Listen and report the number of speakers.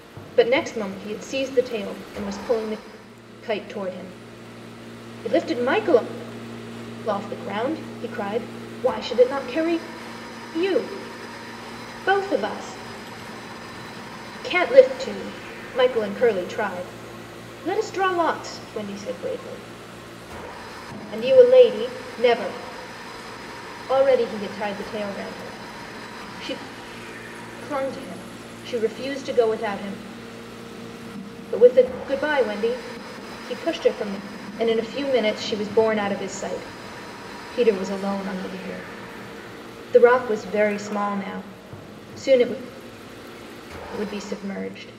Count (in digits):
1